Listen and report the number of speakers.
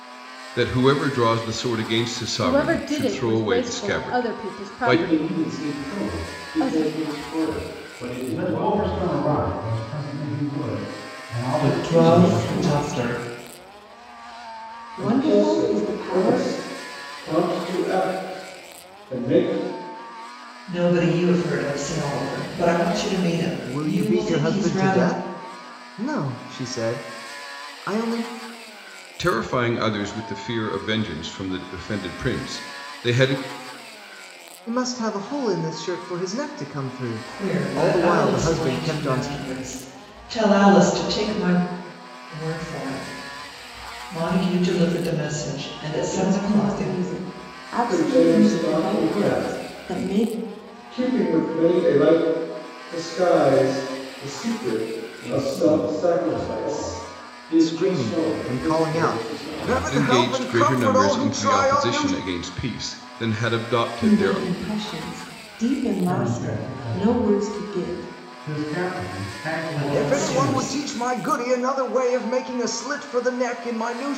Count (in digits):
9